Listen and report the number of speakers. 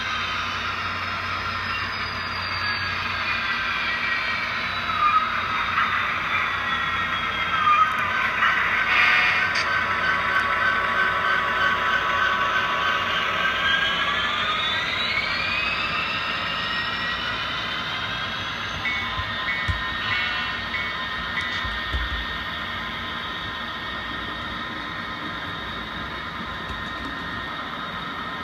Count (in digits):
0